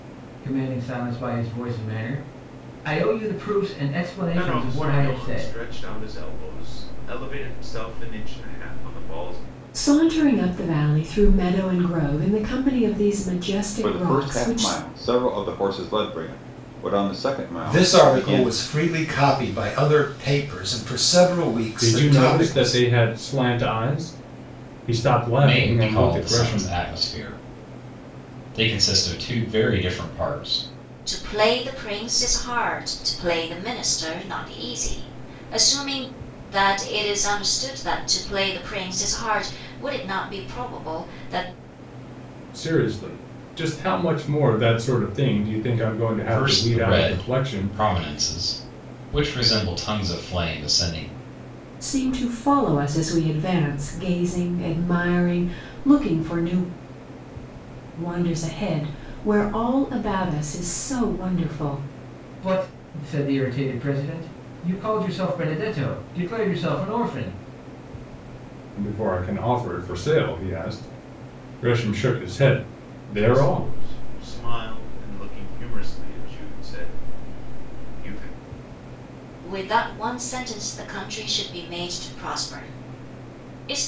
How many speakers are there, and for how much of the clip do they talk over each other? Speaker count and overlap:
eight, about 9%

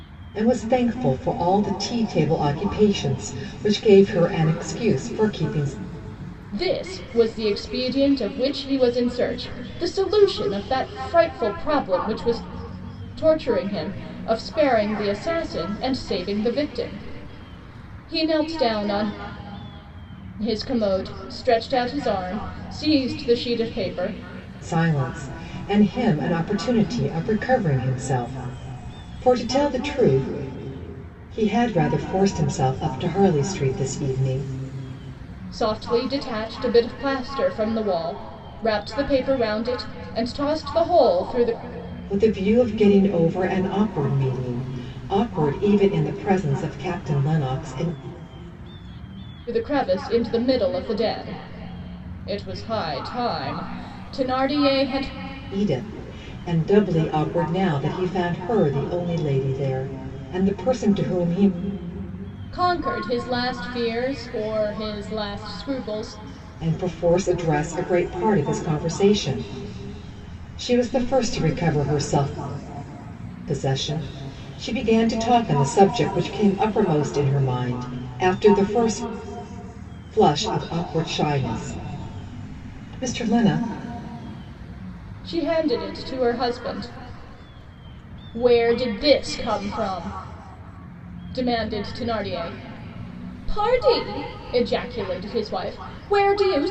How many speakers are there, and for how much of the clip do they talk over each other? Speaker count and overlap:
two, no overlap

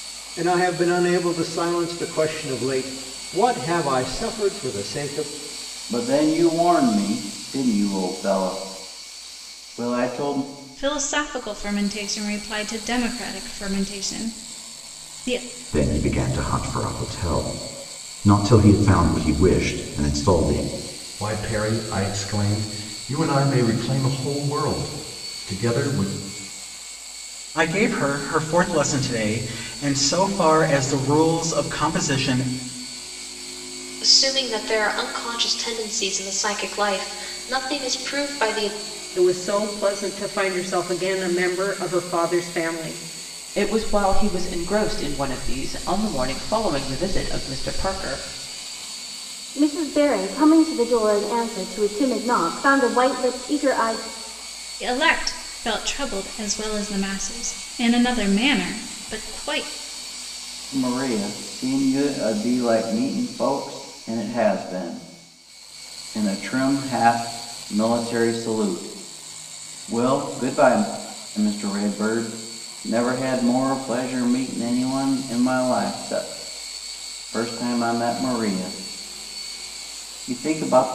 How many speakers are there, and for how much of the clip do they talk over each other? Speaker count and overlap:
ten, no overlap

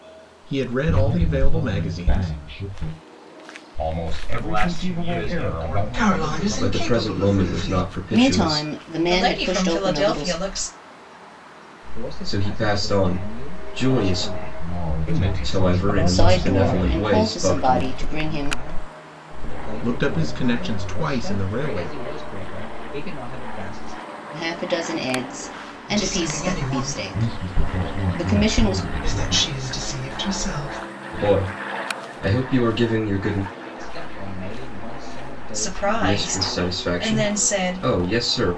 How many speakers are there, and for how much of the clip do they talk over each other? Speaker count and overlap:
nine, about 55%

